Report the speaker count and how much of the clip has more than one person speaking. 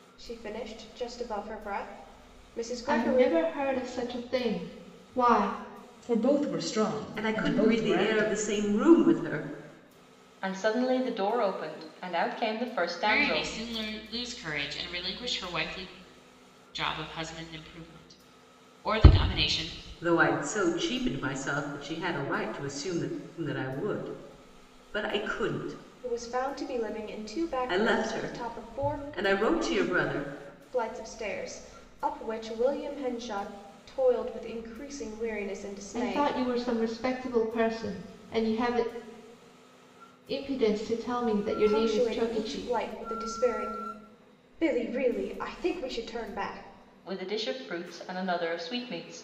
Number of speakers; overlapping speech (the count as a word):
six, about 10%